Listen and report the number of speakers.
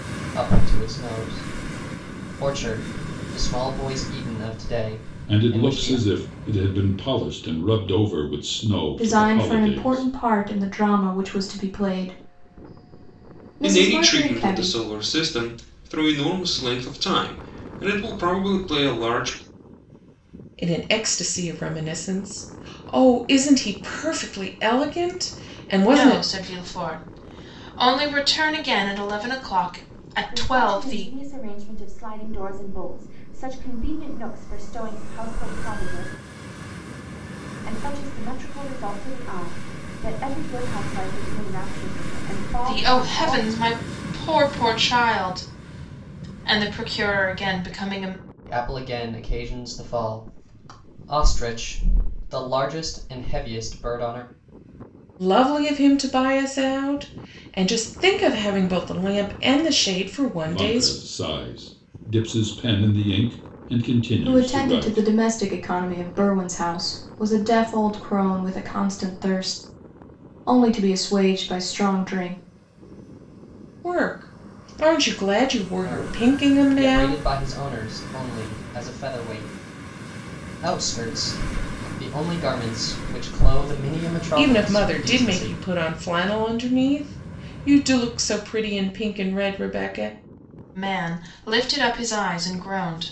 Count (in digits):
7